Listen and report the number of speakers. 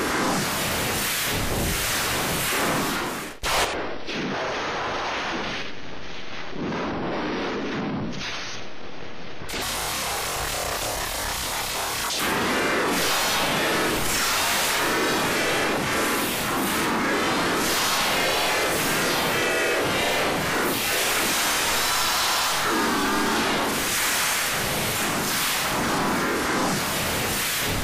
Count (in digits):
0